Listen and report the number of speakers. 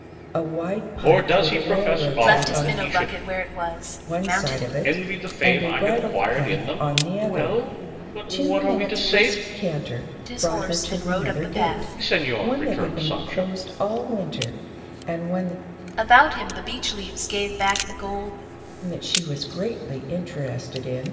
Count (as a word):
three